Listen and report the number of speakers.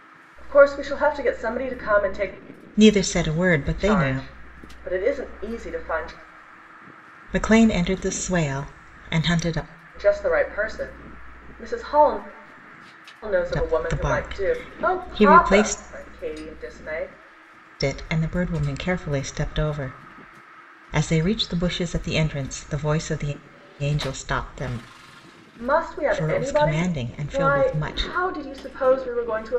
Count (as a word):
two